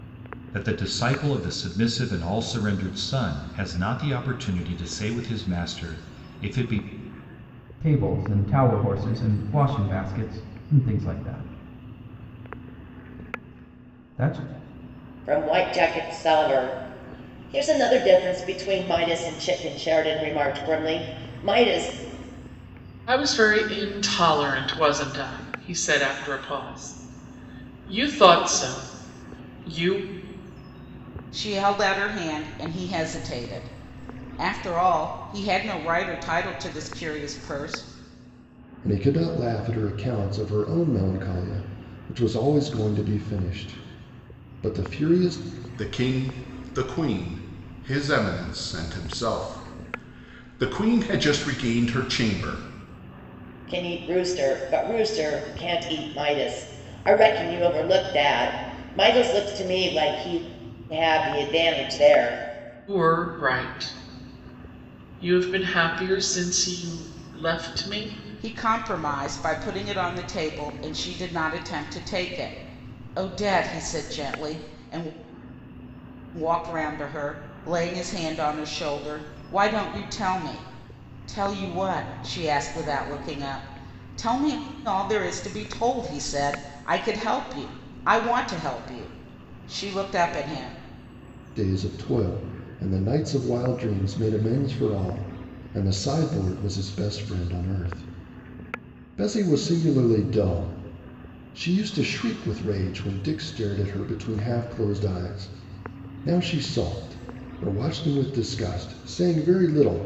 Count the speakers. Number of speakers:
7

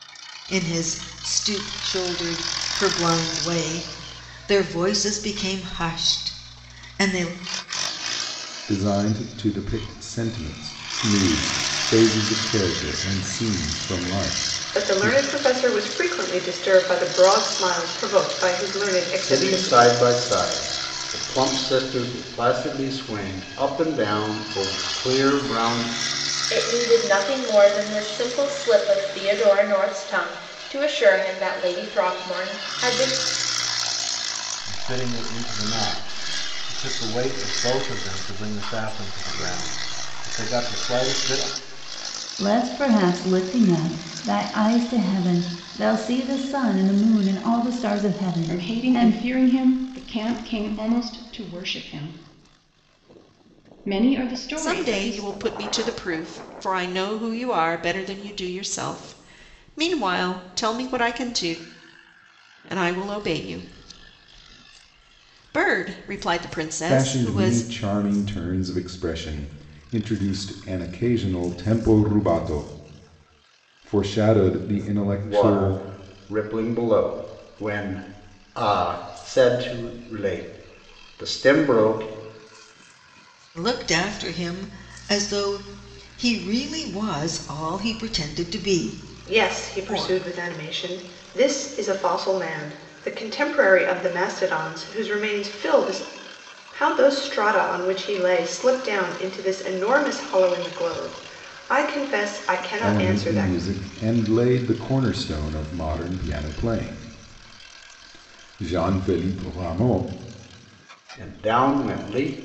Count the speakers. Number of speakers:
9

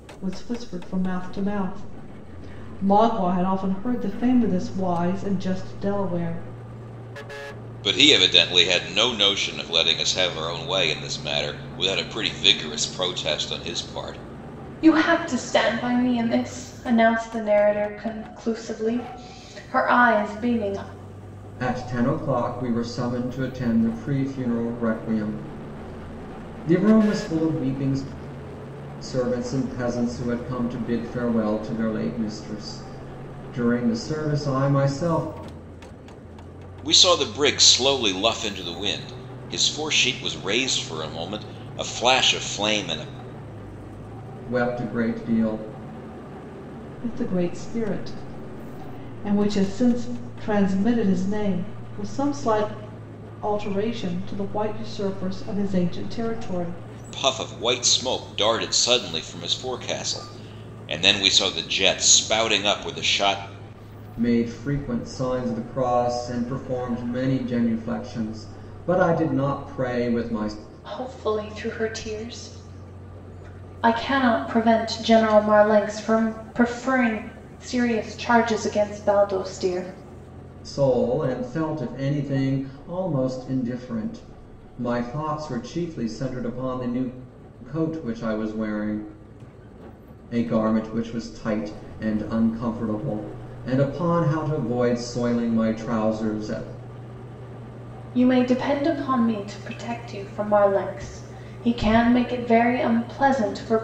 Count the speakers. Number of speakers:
4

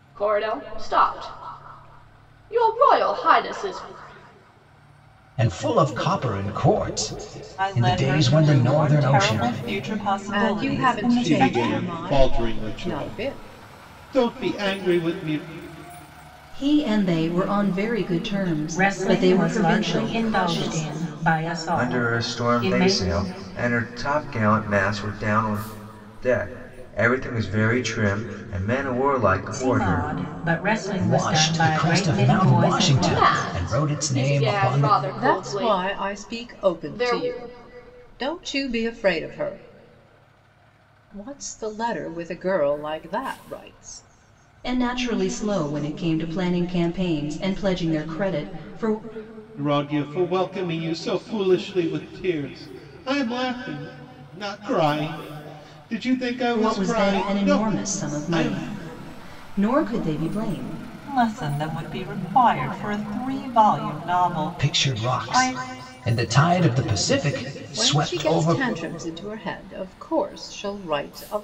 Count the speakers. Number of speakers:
8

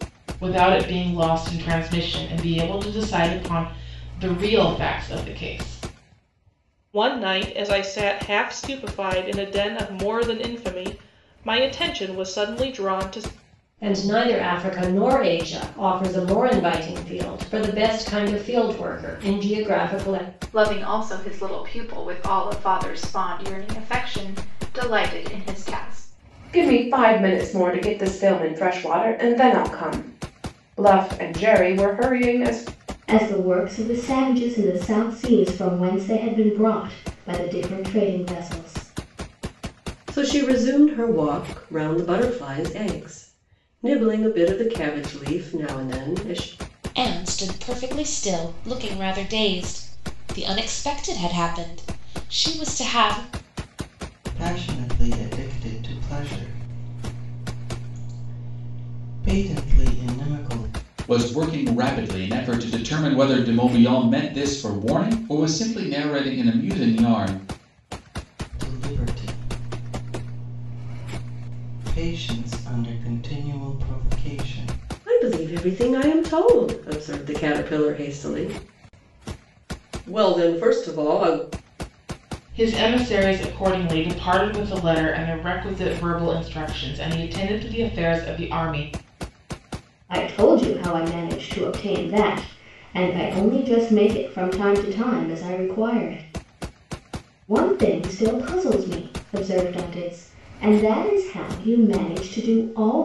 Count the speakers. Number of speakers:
10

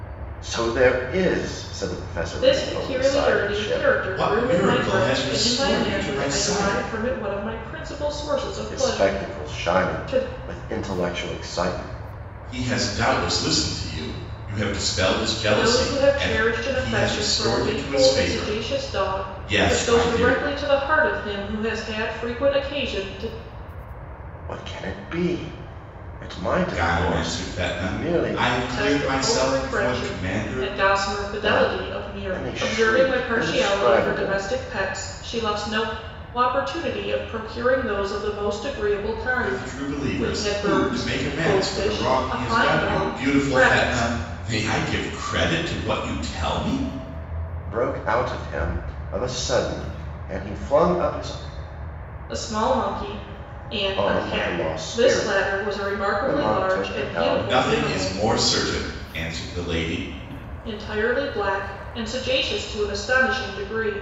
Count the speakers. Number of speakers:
3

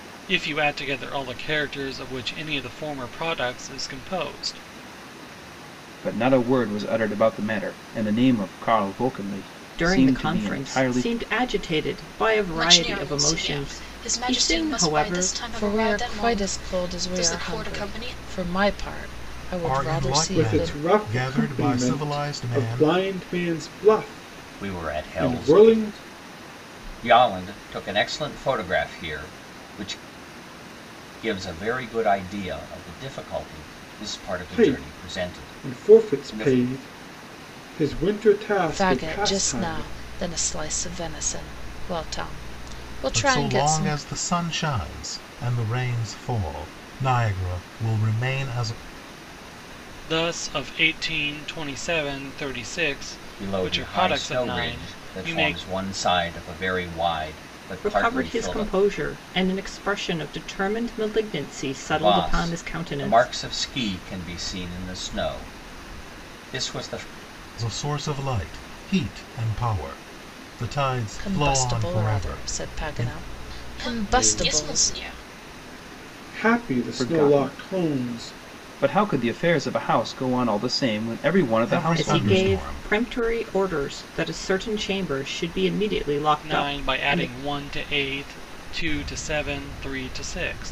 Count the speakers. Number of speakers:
8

